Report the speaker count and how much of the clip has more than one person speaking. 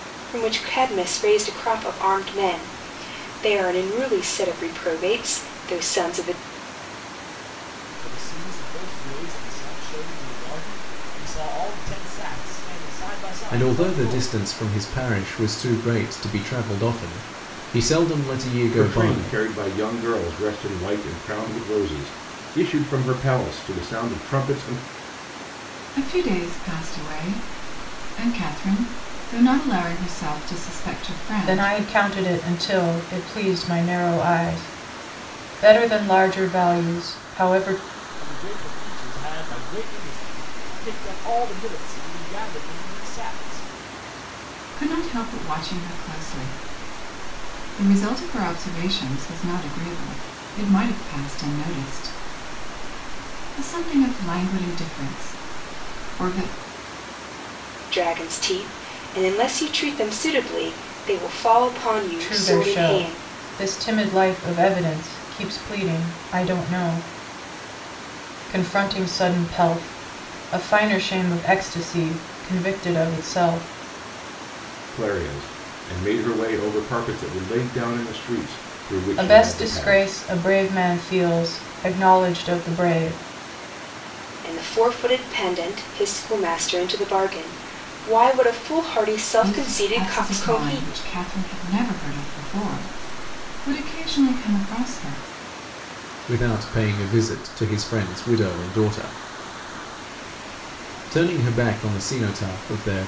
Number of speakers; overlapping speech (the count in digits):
6, about 5%